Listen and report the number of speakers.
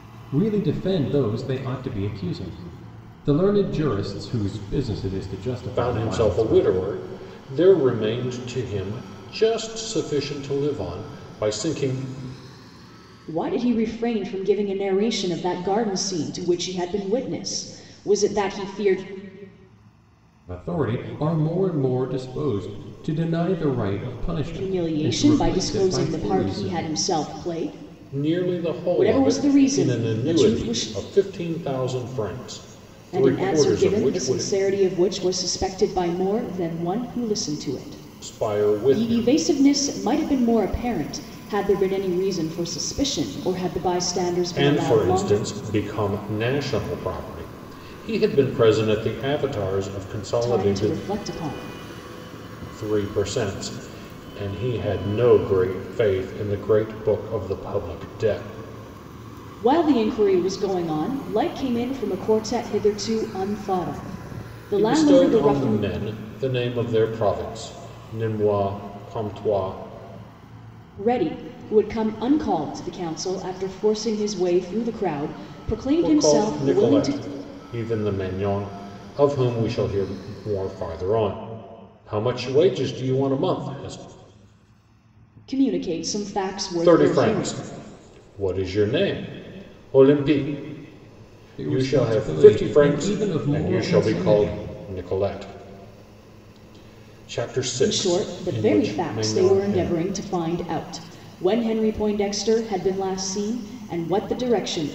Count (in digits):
3